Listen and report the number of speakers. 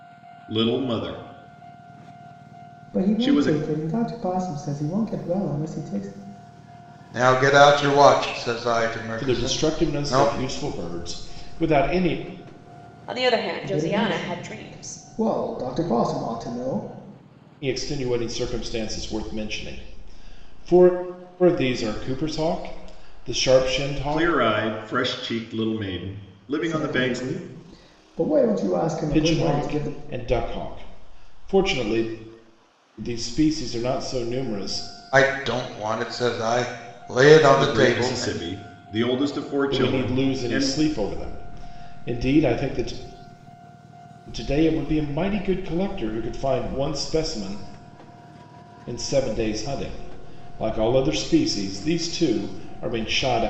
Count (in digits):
5